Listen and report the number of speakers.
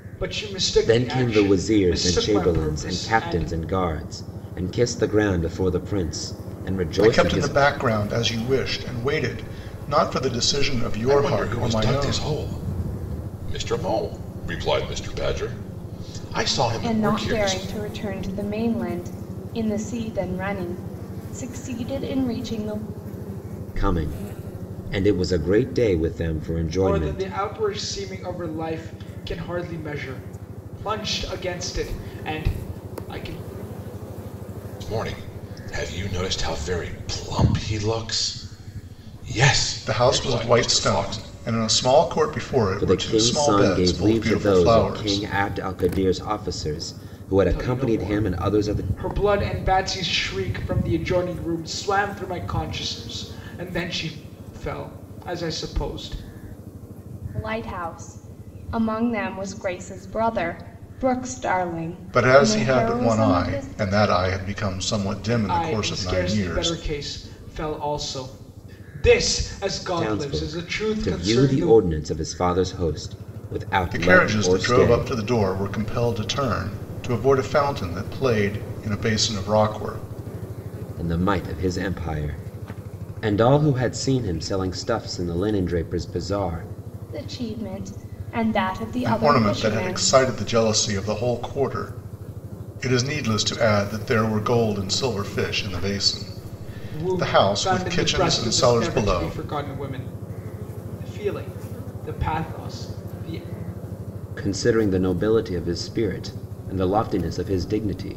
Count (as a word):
five